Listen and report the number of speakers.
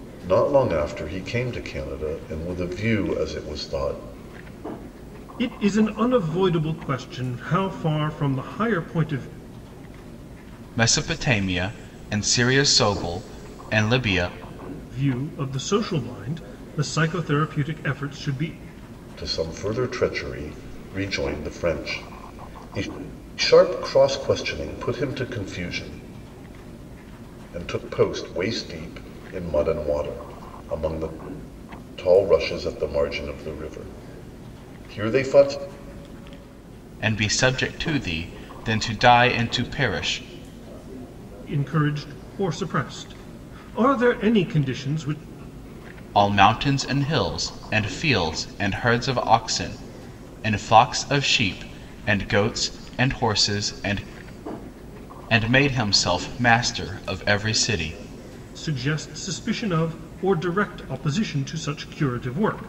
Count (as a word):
three